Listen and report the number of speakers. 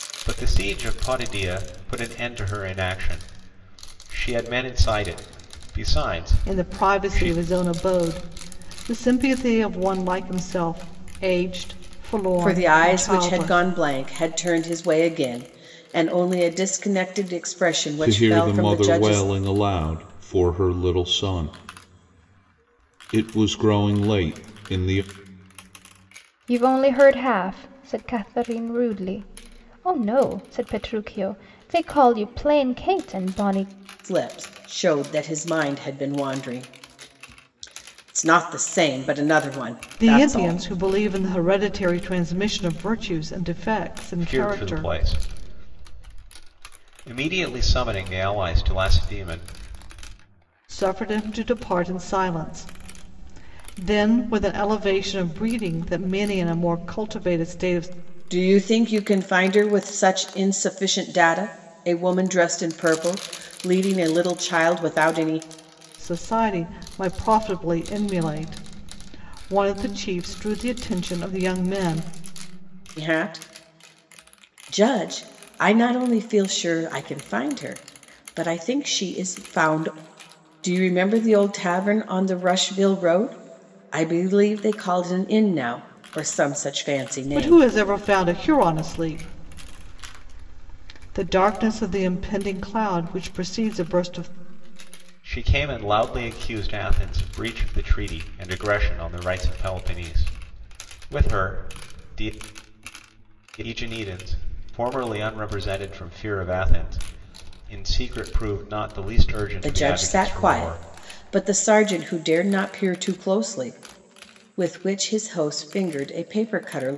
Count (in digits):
5